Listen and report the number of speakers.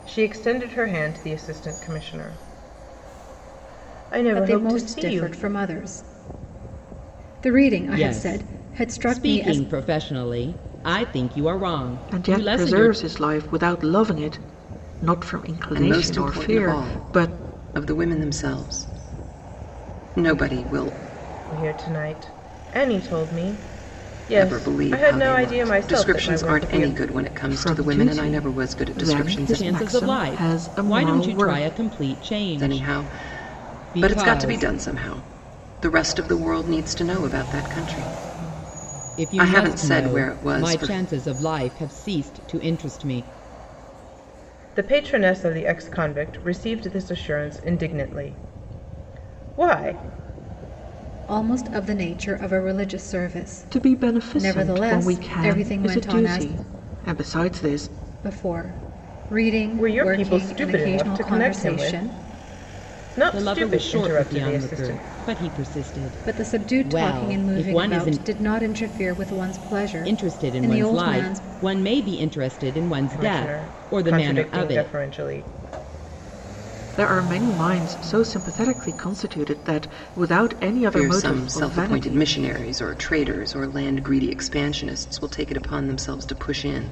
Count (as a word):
five